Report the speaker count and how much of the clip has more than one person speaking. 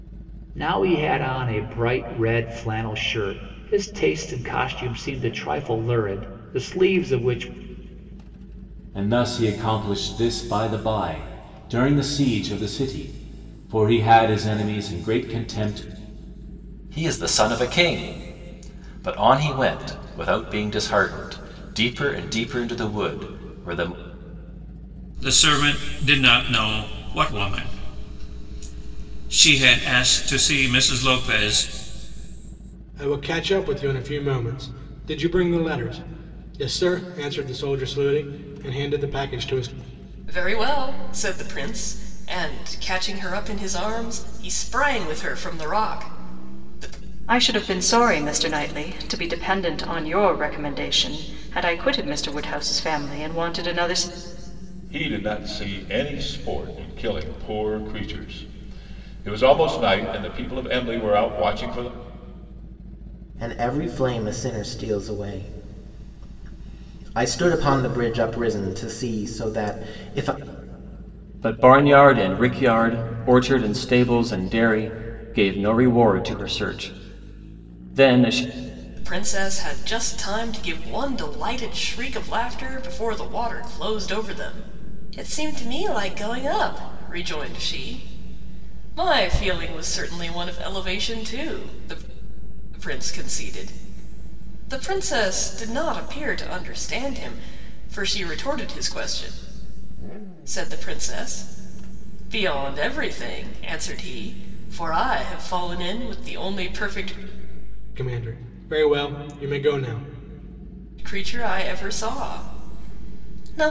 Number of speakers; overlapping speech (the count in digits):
10, no overlap